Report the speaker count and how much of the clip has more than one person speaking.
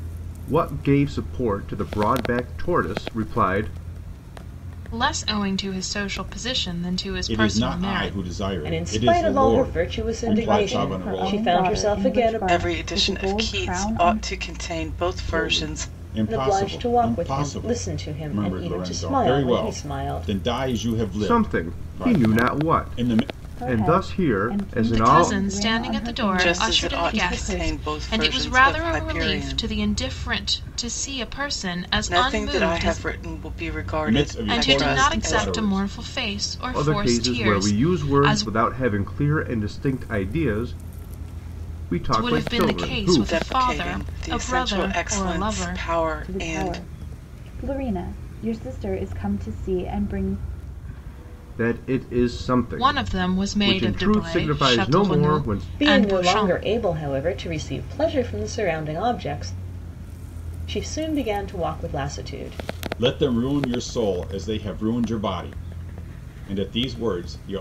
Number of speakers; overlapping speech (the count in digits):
6, about 48%